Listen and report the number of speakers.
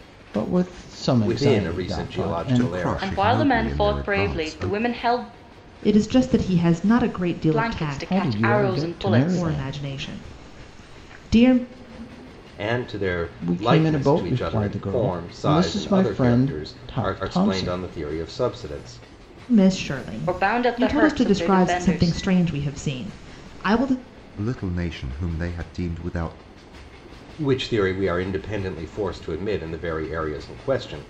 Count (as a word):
five